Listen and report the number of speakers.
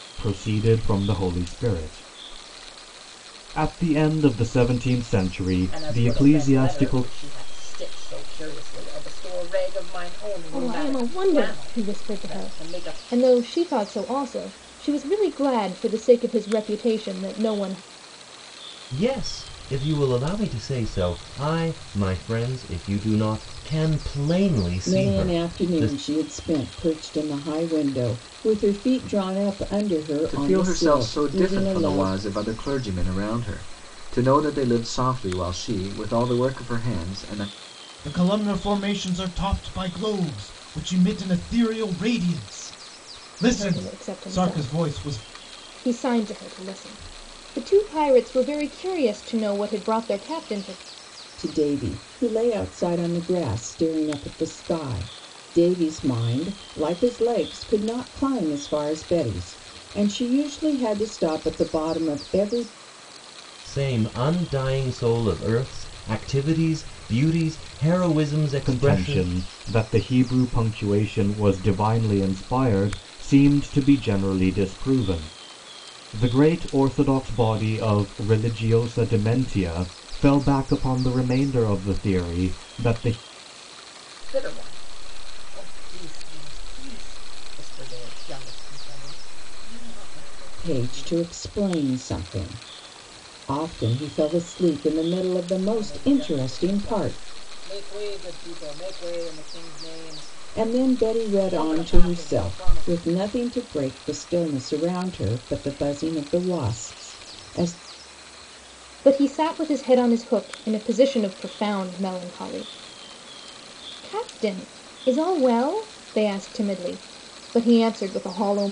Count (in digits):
7